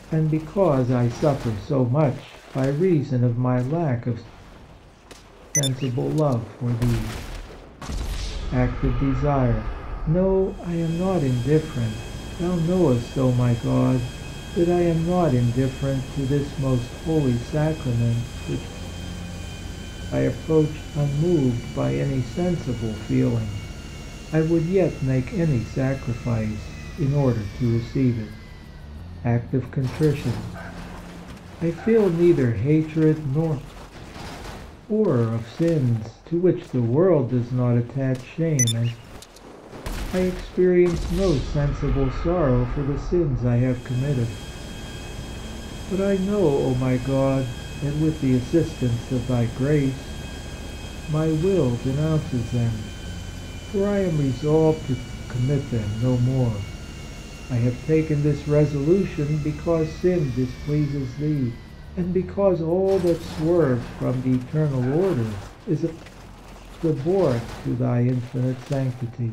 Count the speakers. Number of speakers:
1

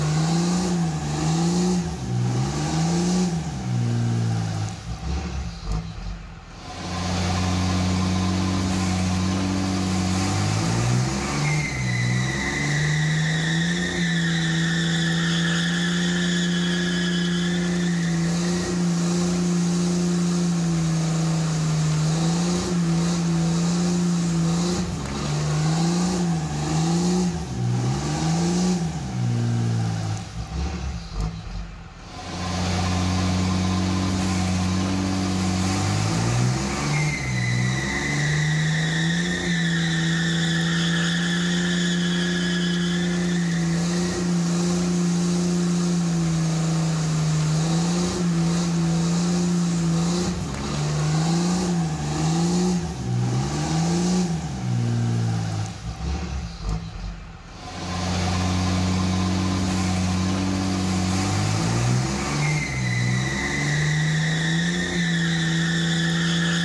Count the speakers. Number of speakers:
0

